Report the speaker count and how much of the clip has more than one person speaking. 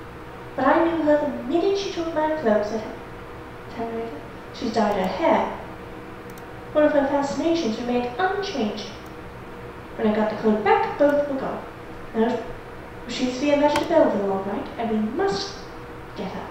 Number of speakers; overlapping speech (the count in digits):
1, no overlap